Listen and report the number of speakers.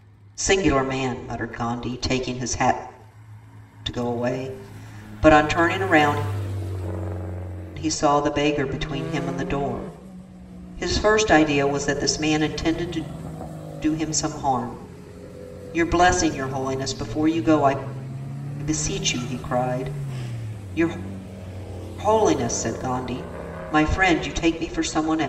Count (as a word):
one